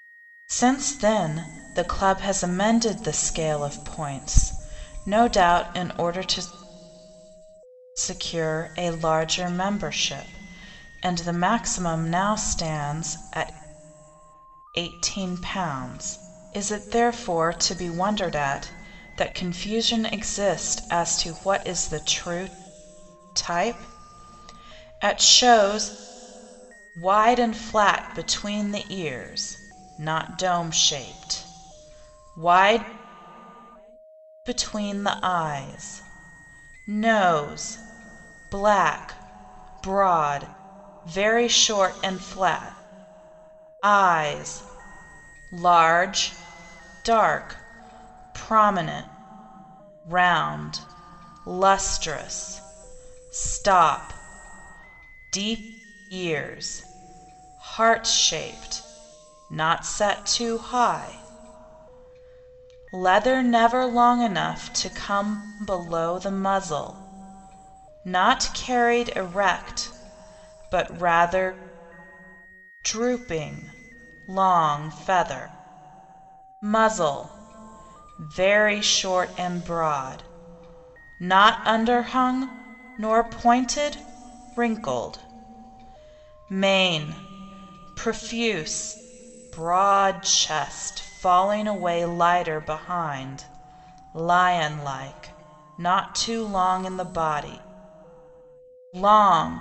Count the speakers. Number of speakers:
1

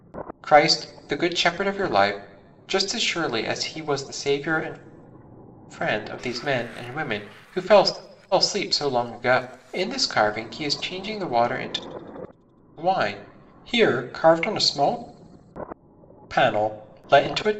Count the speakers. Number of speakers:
1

